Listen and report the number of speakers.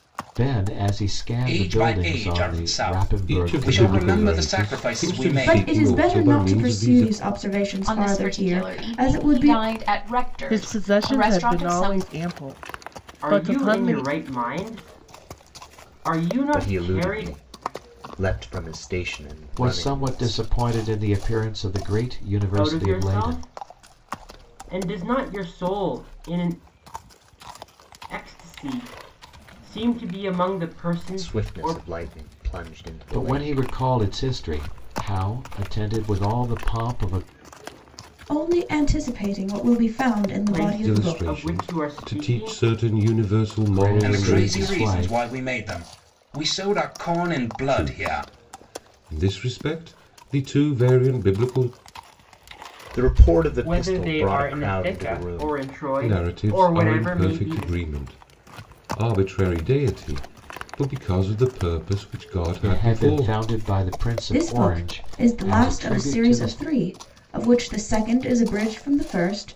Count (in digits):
8